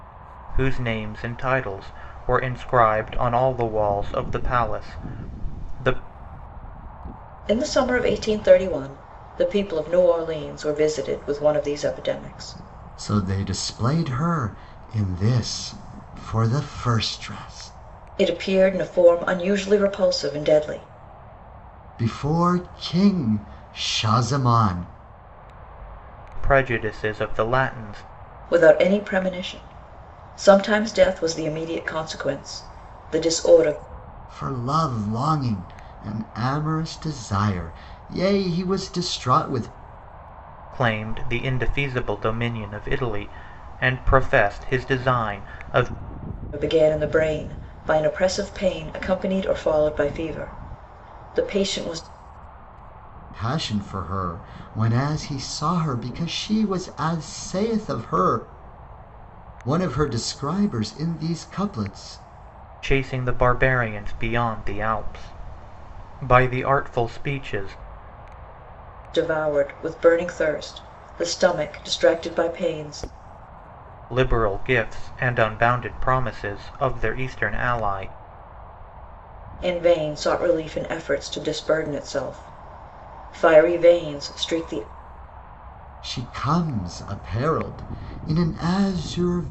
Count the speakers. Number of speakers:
3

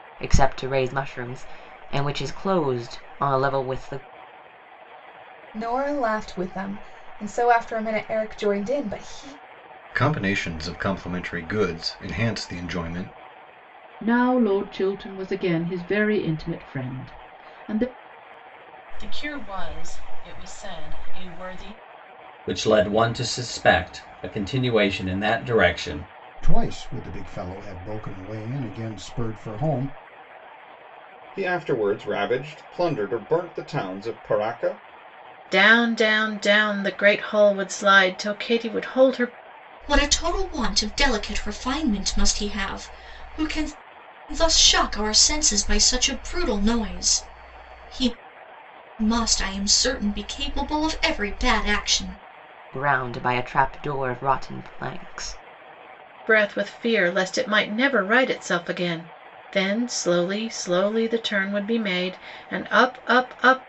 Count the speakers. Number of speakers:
10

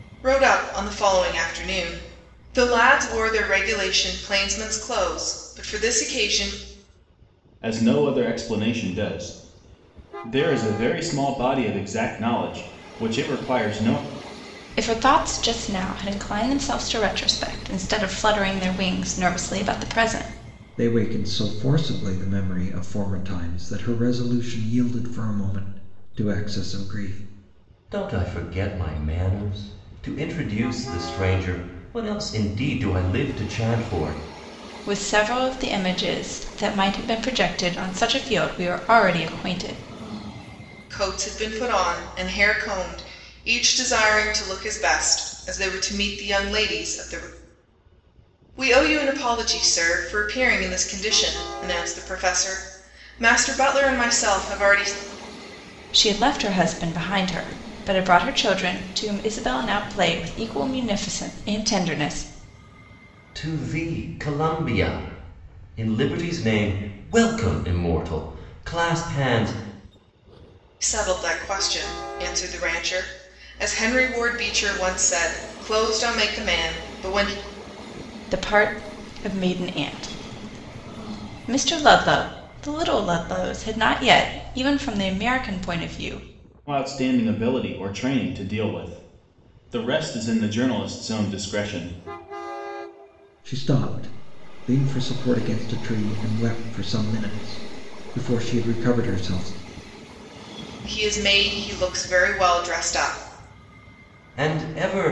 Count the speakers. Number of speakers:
5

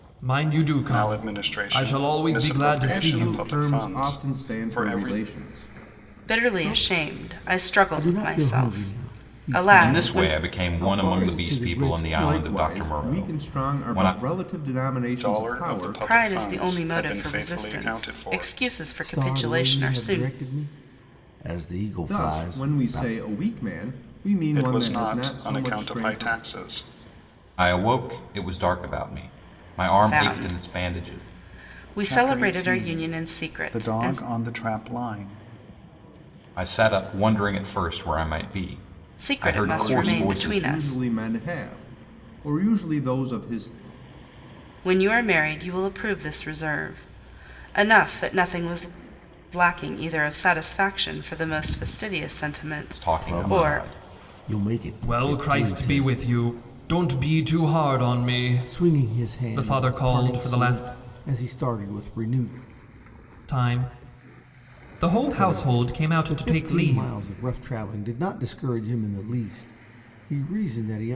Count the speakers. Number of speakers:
6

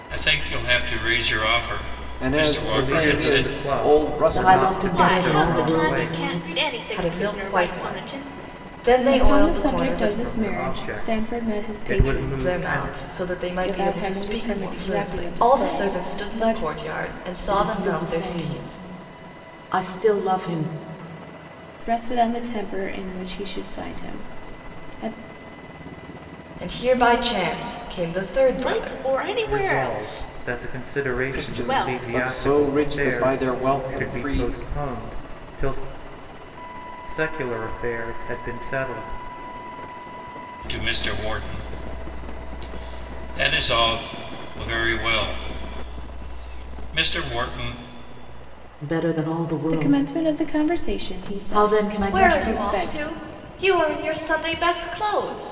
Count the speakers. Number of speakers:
7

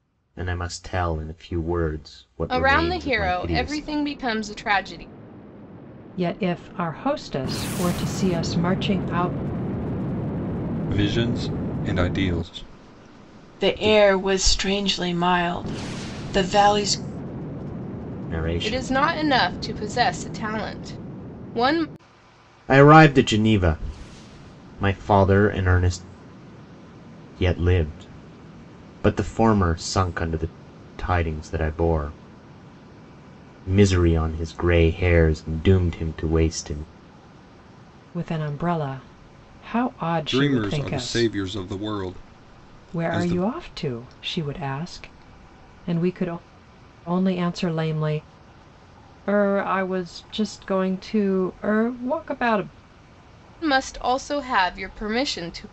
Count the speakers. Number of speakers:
5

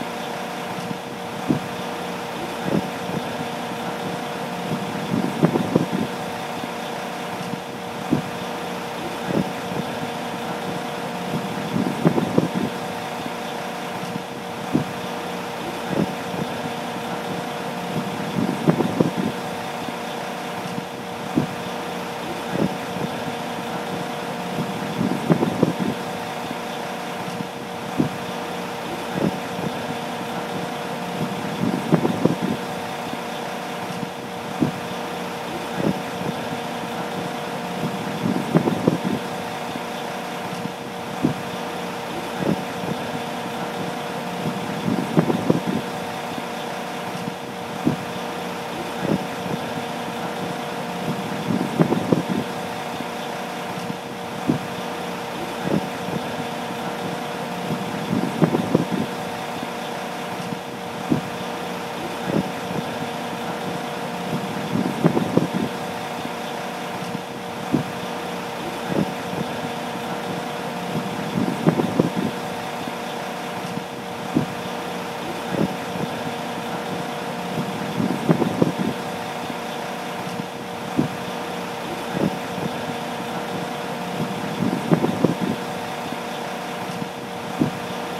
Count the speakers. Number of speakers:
0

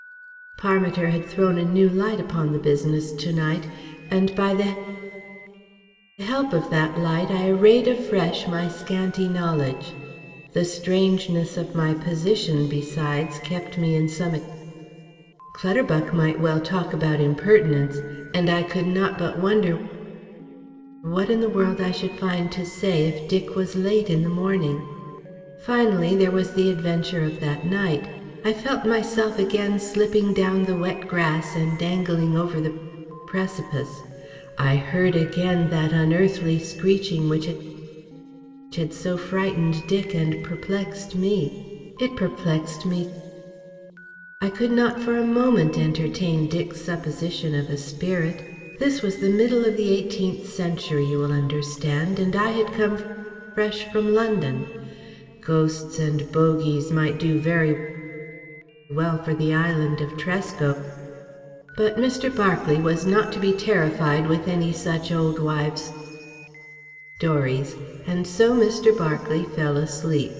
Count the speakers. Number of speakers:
1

